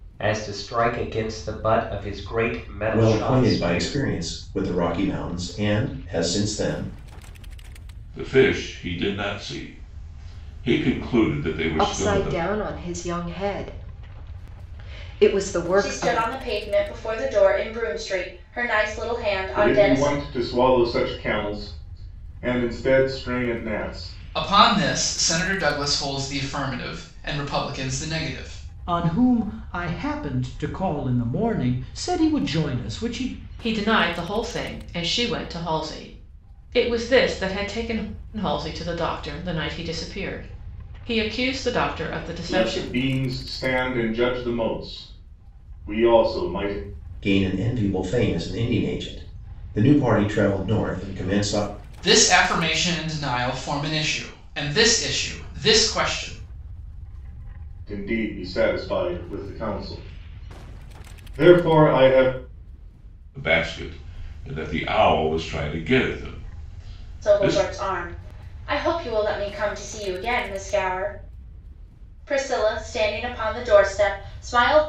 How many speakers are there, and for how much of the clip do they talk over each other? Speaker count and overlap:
9, about 5%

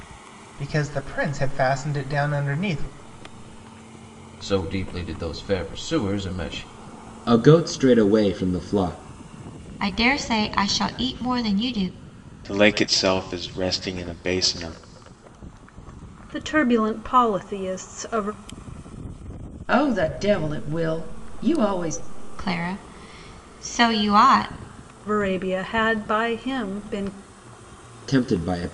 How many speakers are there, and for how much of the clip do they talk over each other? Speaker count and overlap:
7, no overlap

